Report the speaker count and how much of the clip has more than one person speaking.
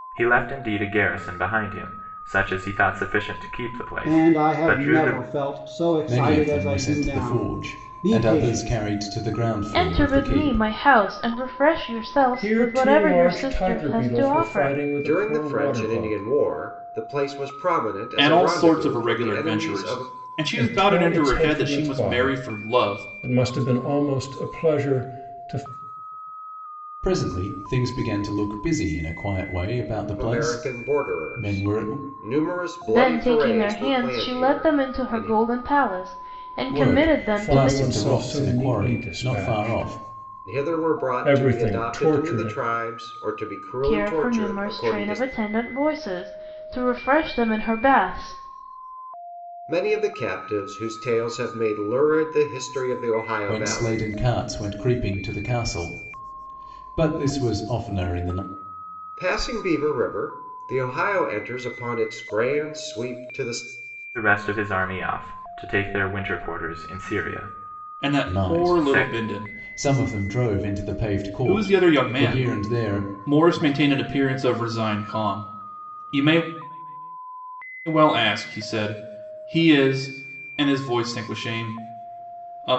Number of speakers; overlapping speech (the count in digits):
7, about 34%